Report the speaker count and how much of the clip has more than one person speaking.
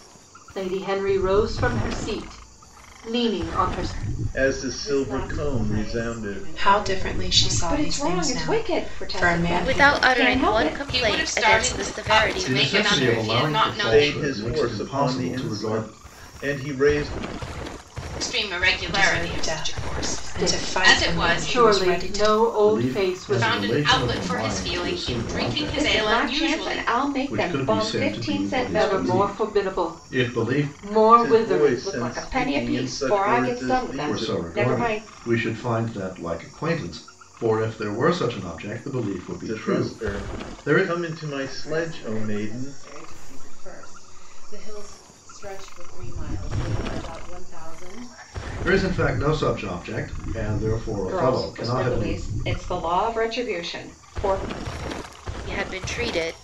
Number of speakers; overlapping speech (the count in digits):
8, about 53%